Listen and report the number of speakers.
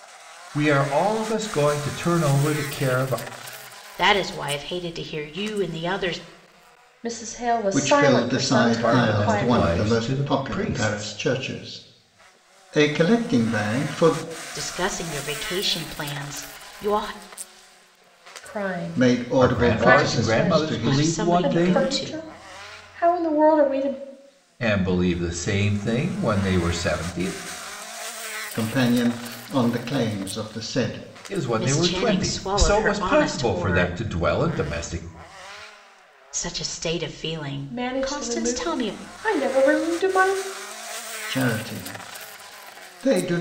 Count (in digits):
4